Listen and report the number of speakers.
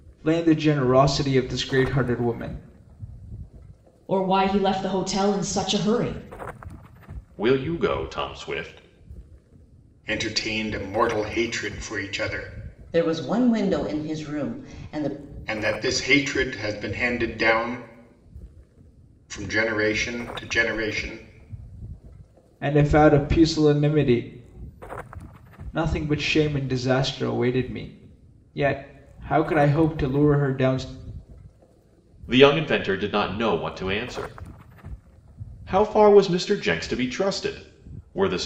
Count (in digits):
5